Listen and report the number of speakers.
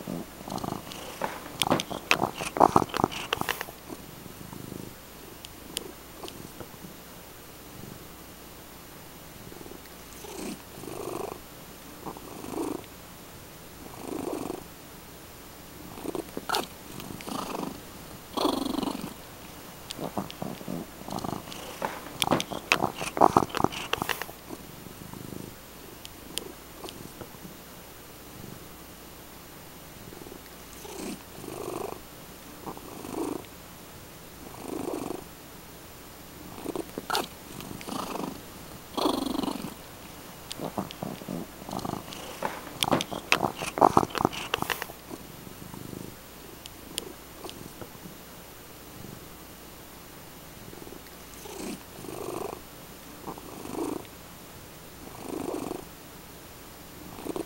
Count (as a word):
zero